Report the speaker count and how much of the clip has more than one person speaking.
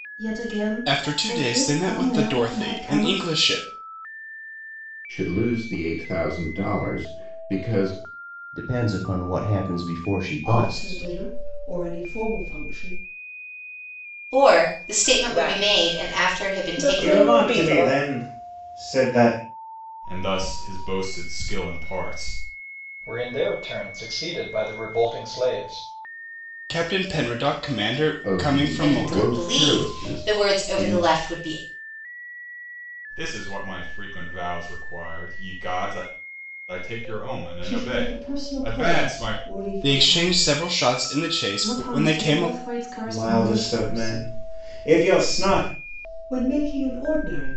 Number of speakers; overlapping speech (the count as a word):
ten, about 31%